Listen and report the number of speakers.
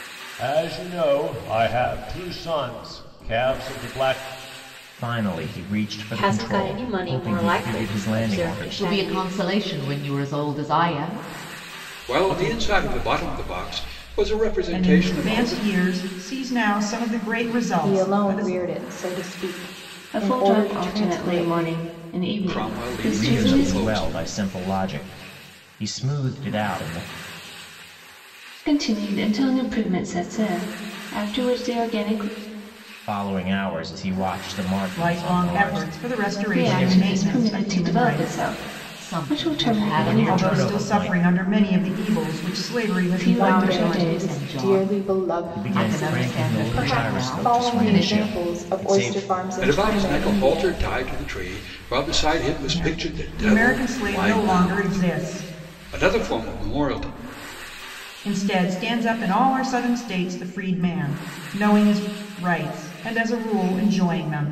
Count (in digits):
8